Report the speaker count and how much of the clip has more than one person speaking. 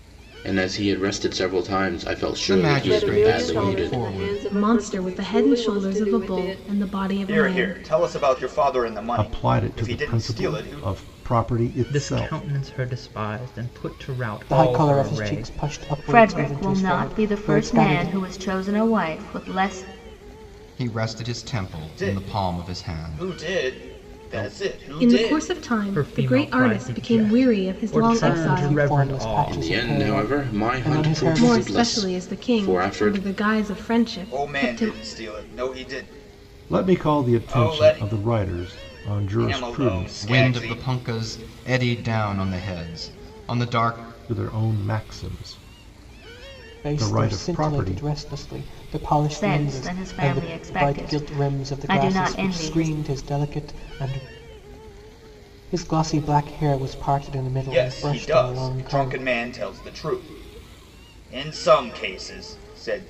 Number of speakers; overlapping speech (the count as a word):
nine, about 49%